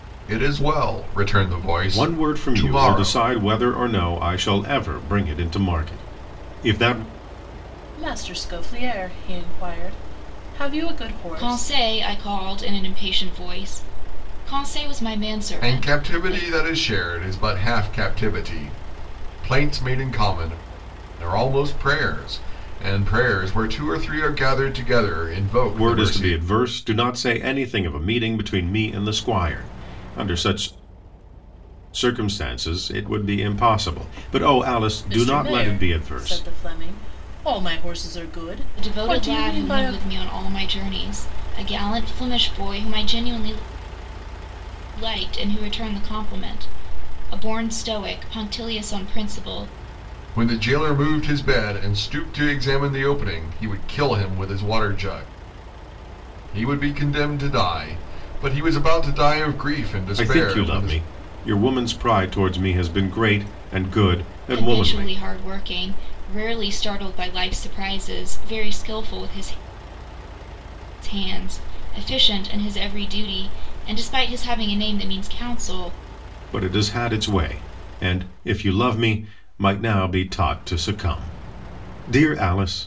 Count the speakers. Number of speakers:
four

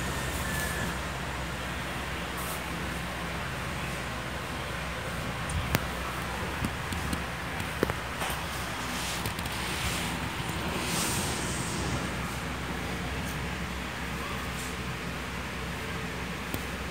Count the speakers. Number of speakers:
zero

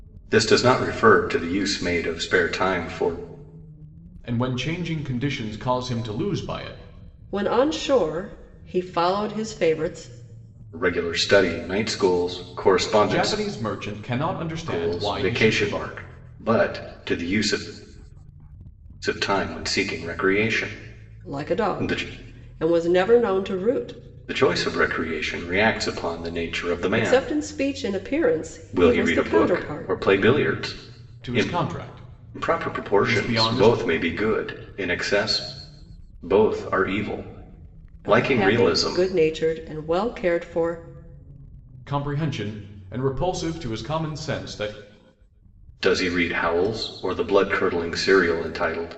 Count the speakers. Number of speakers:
three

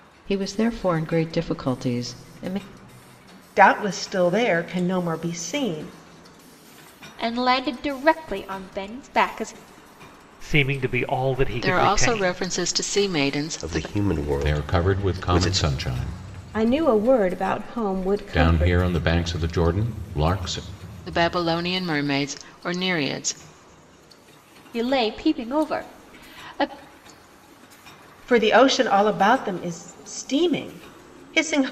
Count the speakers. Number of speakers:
eight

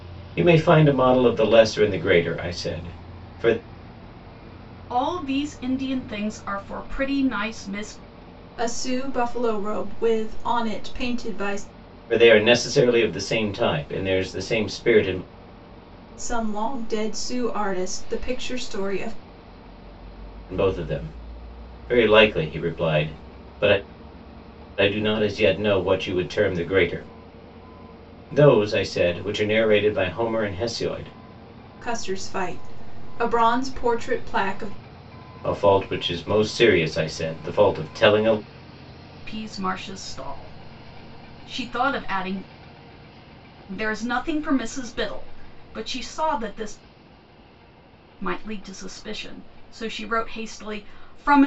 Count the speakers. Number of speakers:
three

